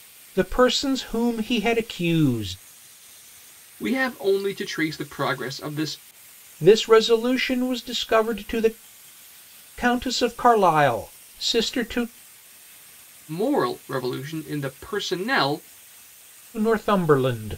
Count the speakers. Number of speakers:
2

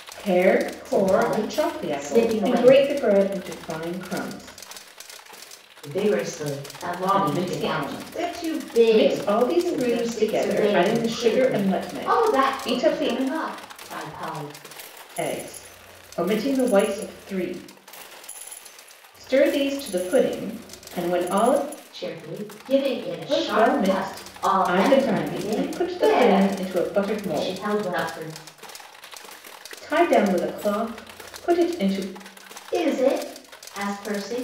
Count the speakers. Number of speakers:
2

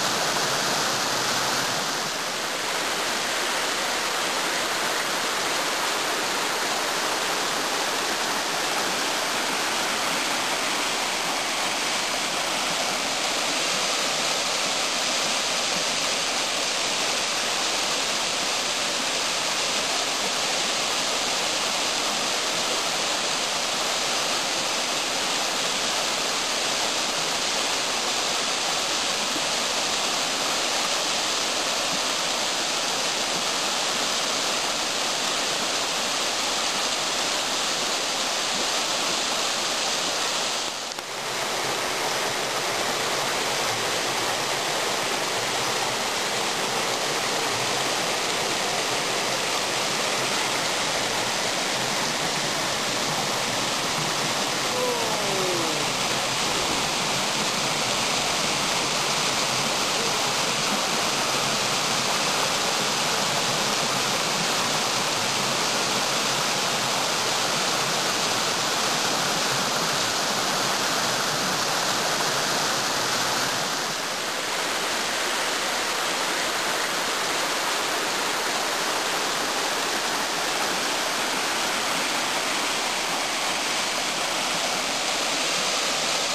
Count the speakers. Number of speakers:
0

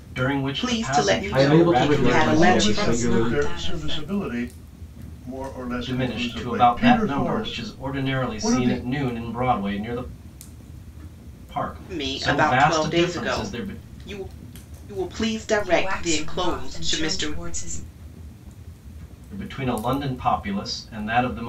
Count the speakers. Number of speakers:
5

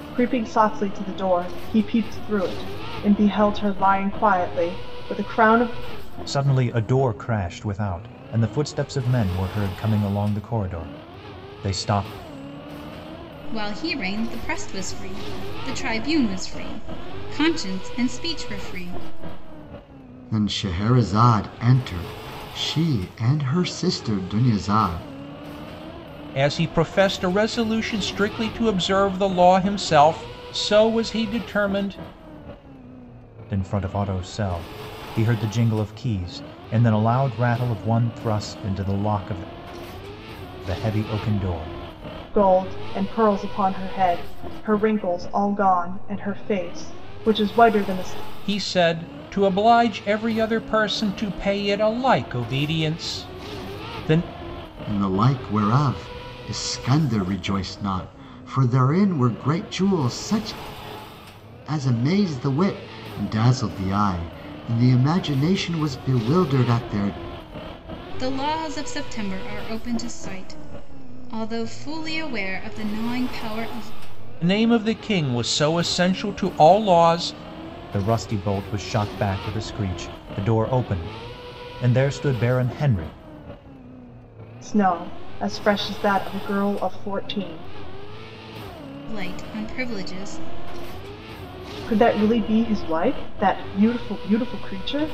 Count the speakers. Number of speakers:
5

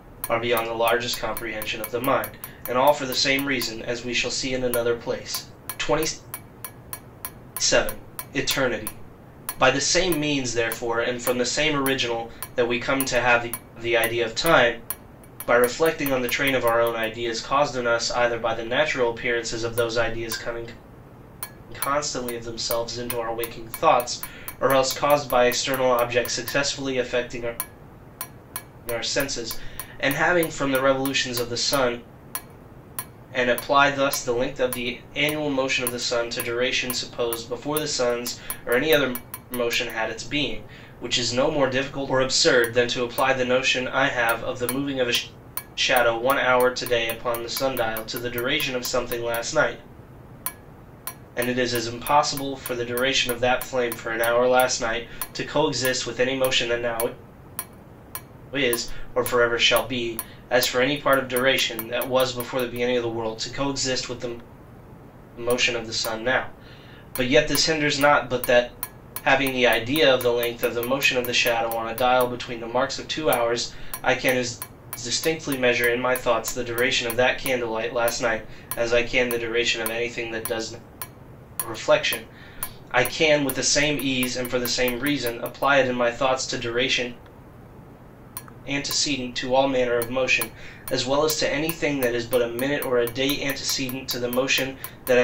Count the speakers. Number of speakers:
1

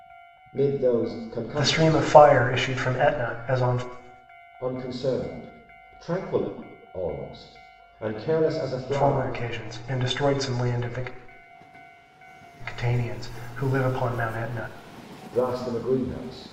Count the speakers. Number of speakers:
2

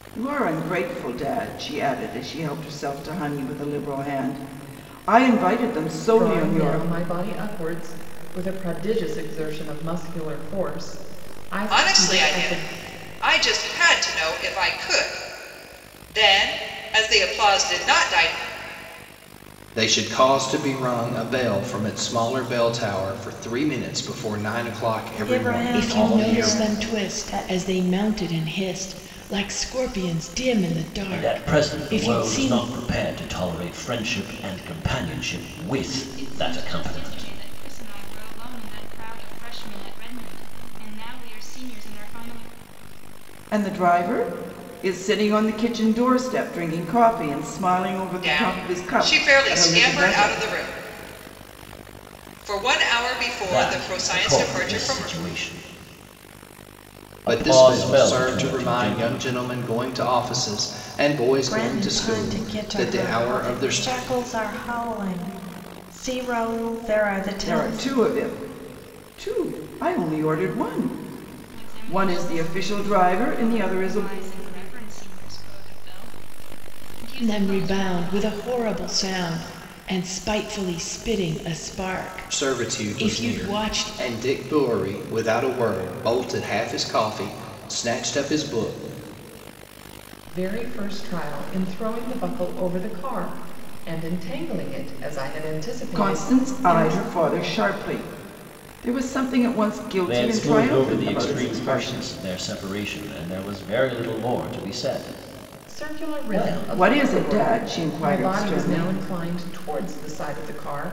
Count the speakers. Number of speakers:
8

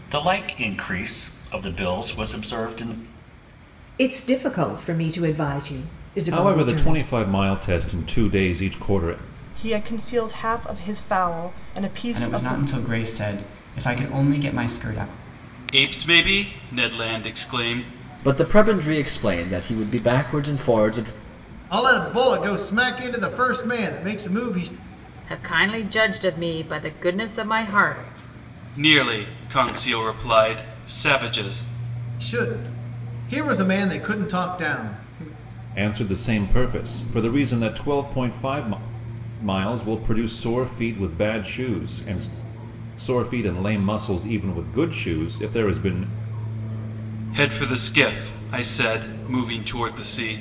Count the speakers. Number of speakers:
9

